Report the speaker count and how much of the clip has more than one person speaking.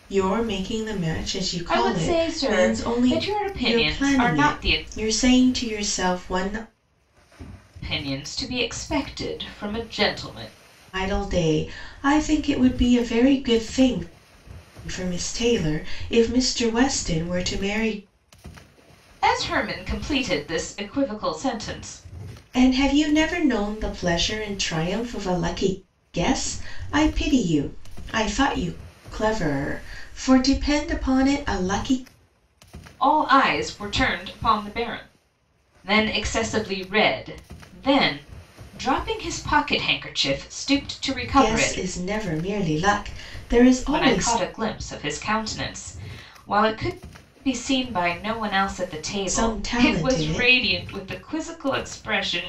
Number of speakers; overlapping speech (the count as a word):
two, about 9%